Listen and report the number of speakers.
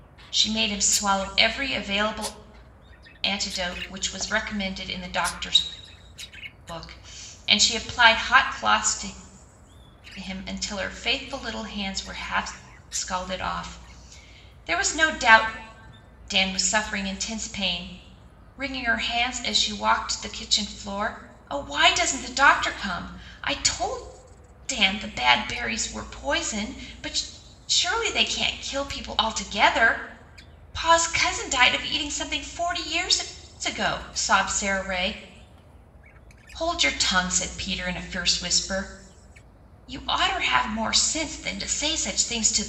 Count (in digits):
1